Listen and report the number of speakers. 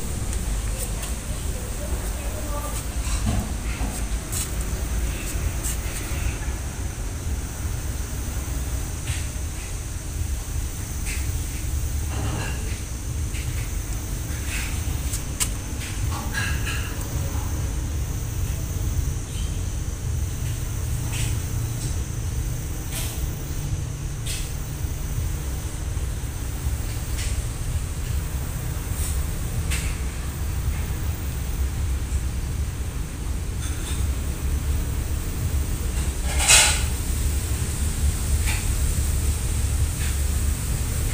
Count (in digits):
0